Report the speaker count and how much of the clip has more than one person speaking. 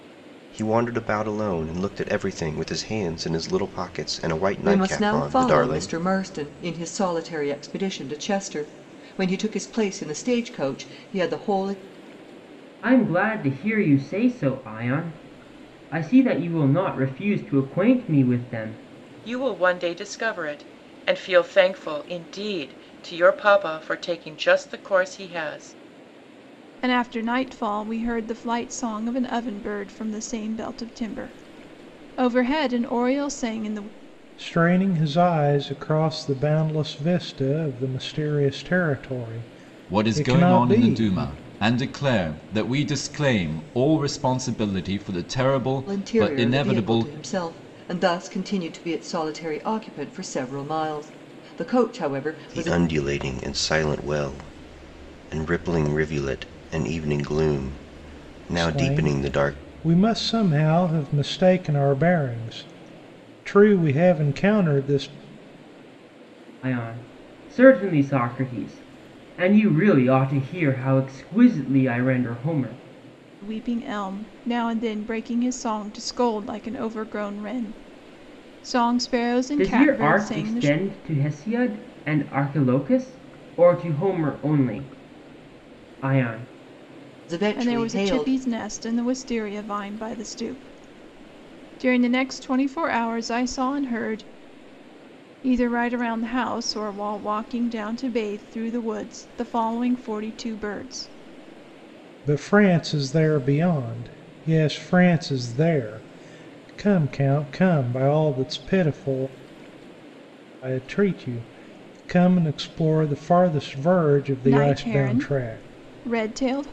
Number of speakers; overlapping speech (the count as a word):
seven, about 8%